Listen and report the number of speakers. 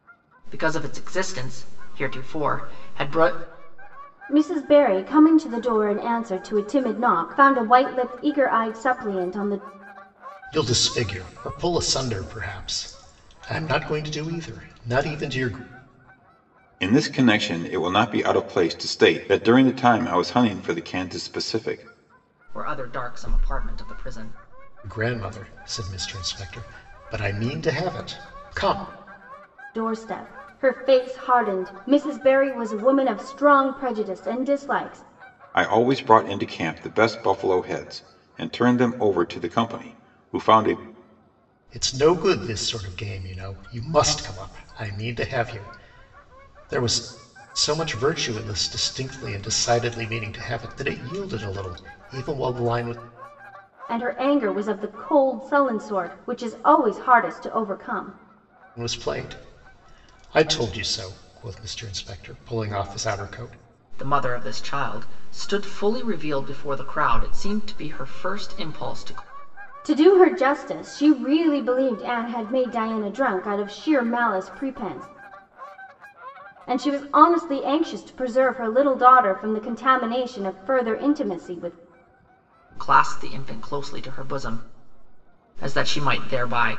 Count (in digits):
4